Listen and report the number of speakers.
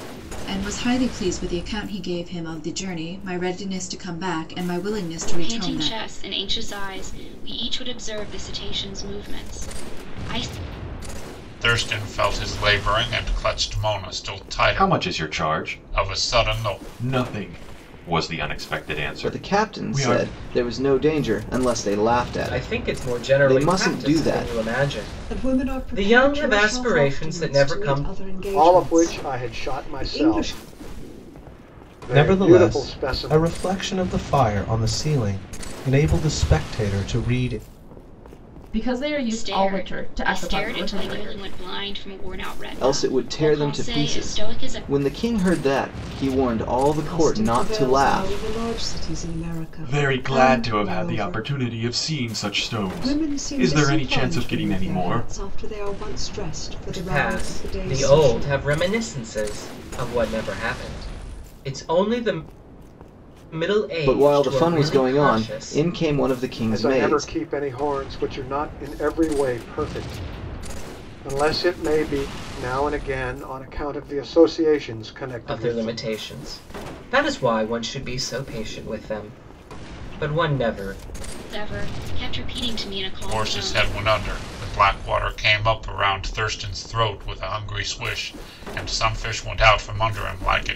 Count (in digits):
10